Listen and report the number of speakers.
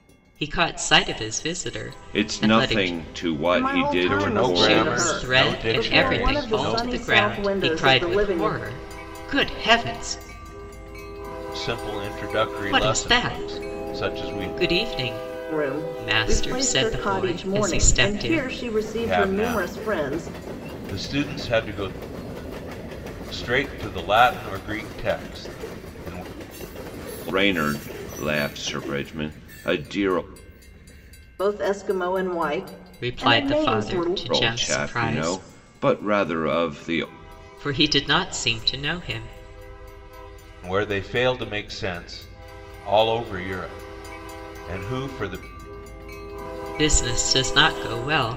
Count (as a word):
four